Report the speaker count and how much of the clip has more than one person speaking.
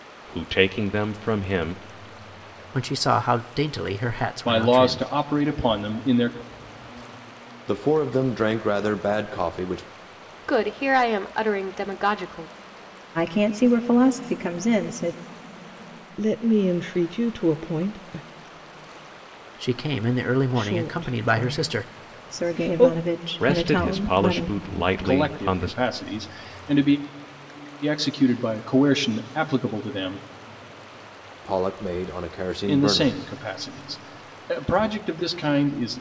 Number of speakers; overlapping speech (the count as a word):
seven, about 15%